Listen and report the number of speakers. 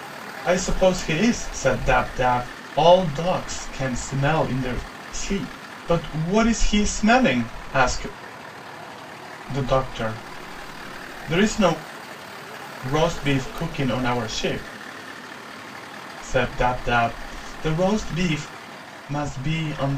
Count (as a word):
one